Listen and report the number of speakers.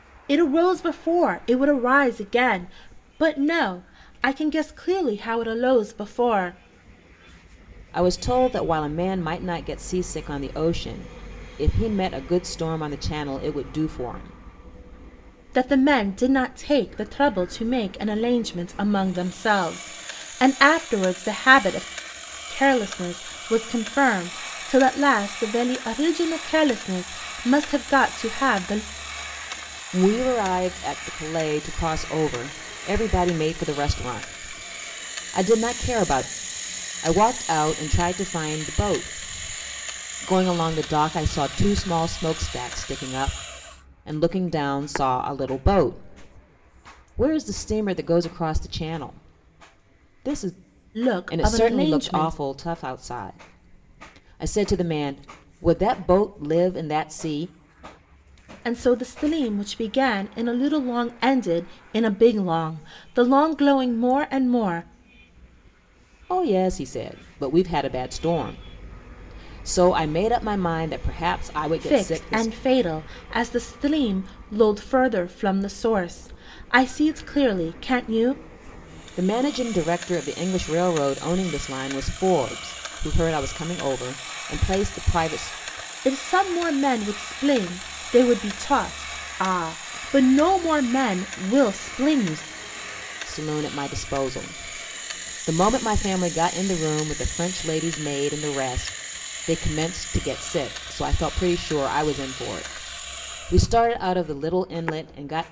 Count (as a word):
two